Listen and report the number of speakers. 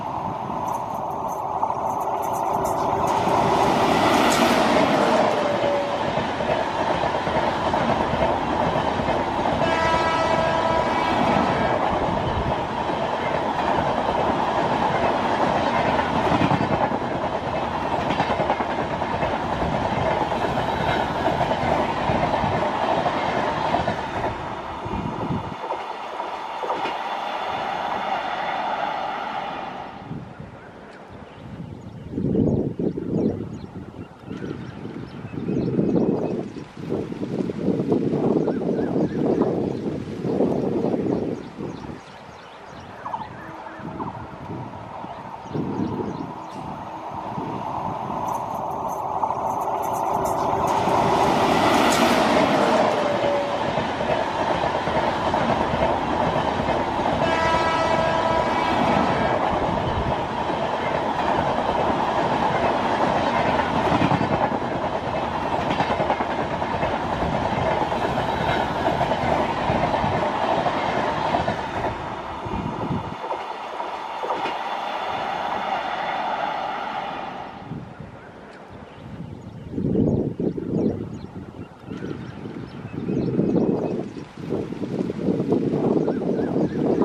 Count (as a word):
zero